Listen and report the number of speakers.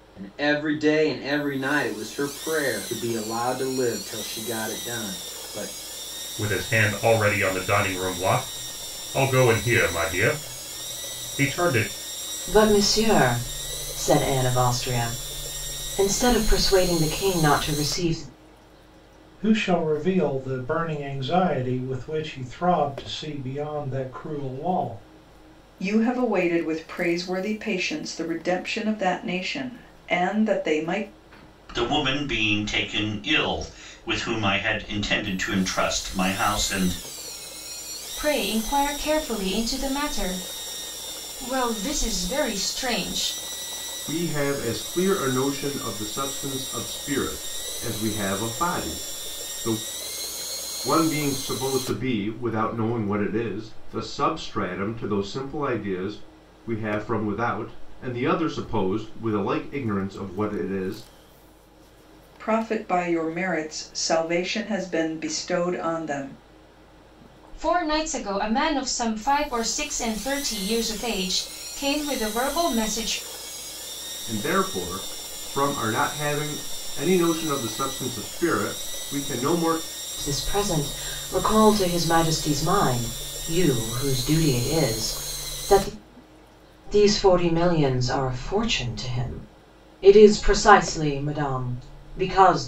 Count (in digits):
8